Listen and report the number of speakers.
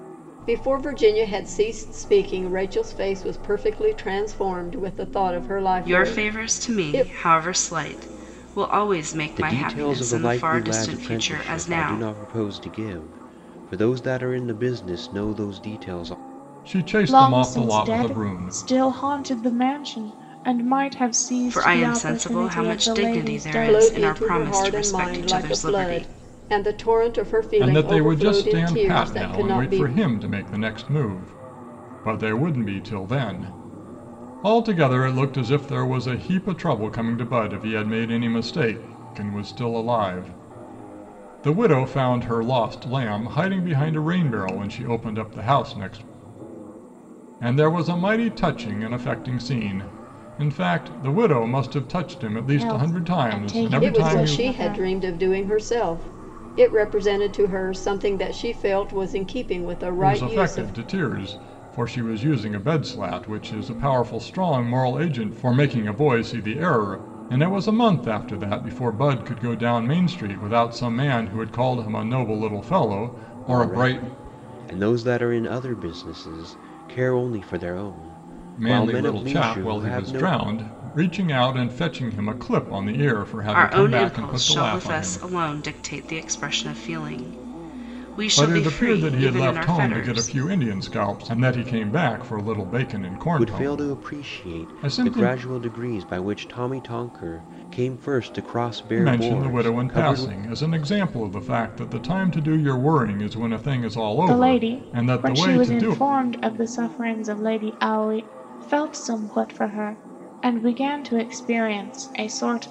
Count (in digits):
5